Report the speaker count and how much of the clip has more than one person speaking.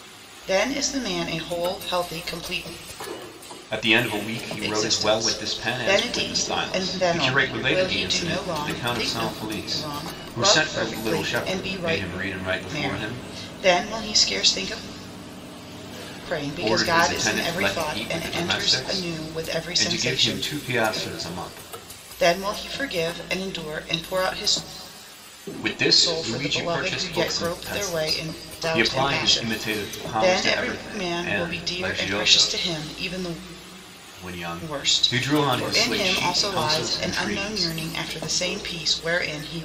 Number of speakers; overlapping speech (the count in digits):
2, about 51%